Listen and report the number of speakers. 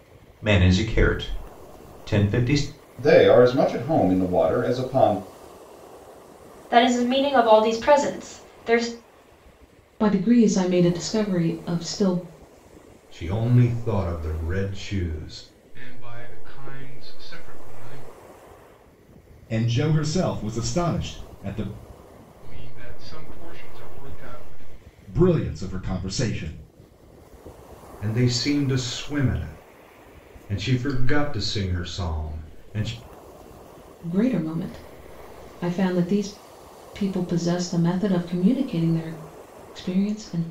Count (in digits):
7